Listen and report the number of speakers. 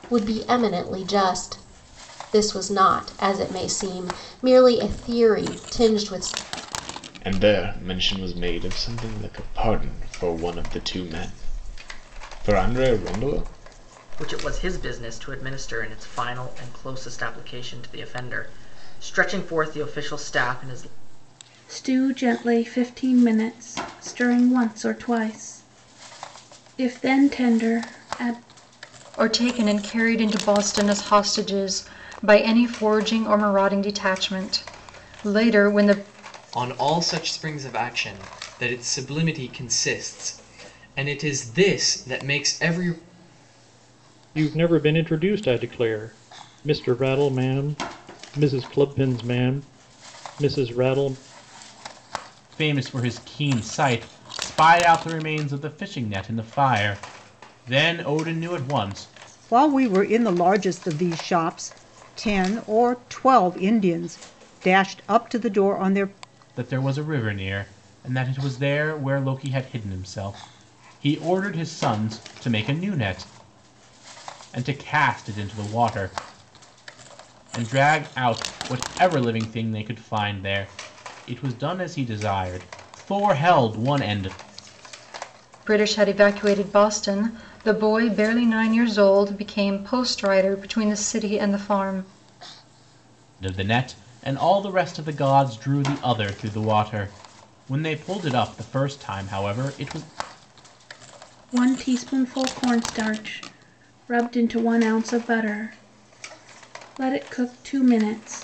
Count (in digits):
9